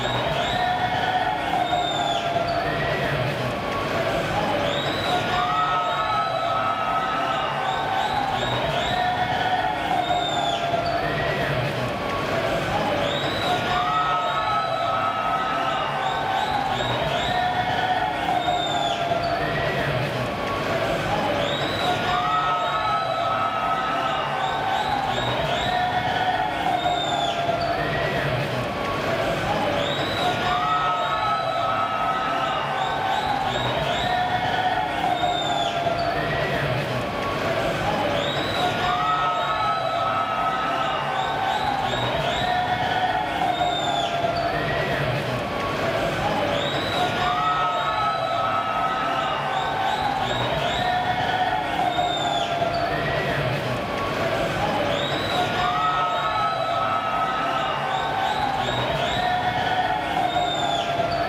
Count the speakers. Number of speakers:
0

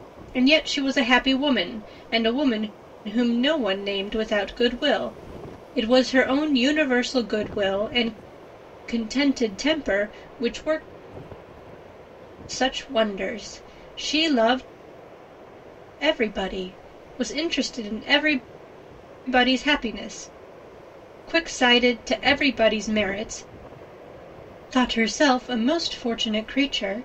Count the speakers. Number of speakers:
1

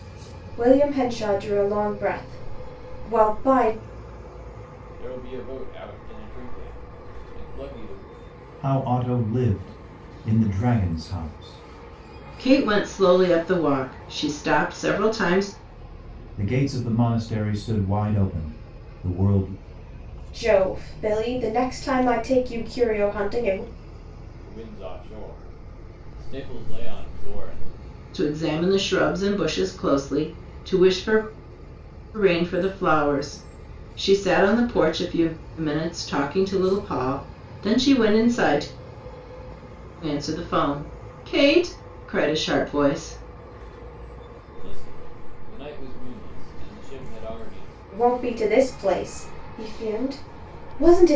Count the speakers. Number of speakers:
4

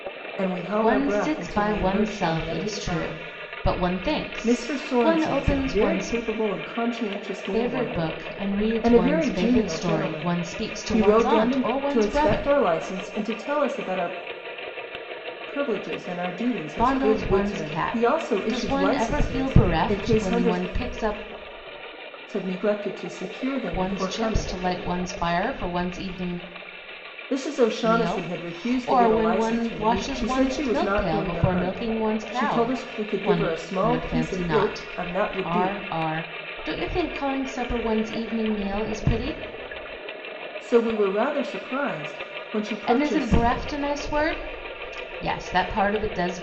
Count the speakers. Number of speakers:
2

